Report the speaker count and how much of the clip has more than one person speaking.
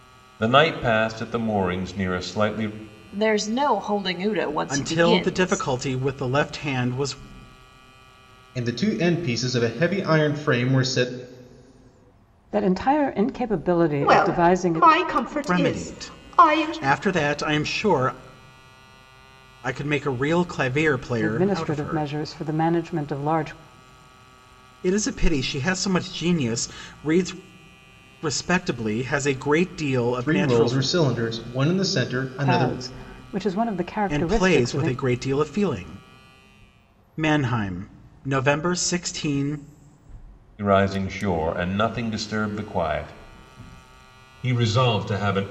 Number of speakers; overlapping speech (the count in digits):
6, about 13%